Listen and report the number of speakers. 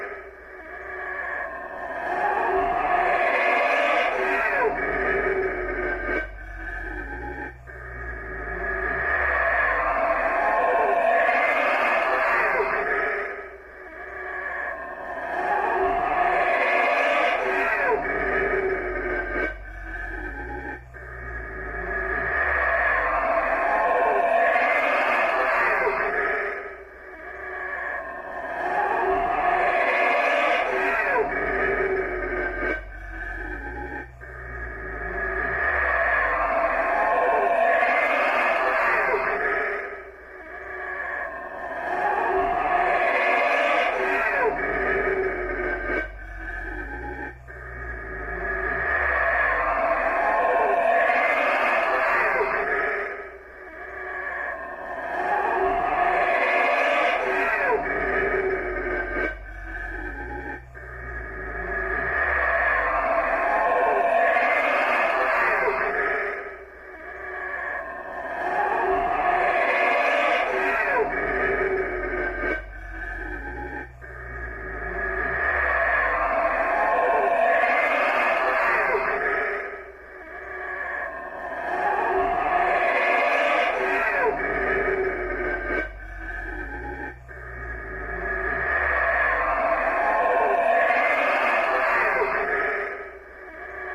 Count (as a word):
zero